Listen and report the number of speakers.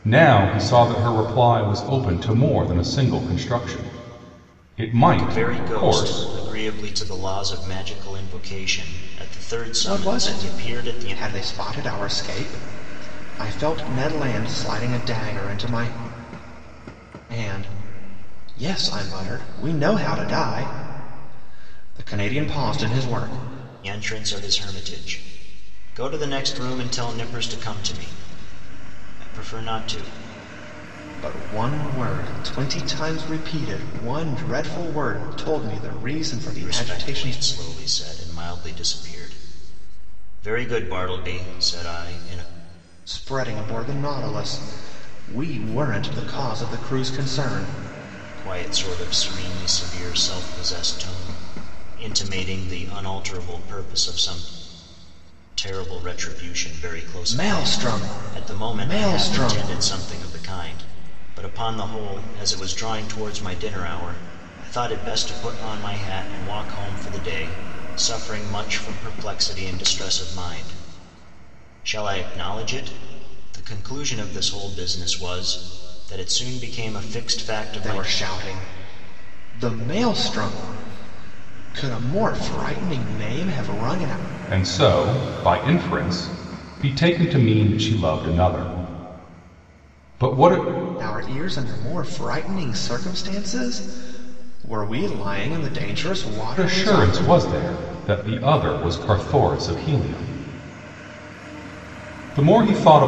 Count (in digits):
3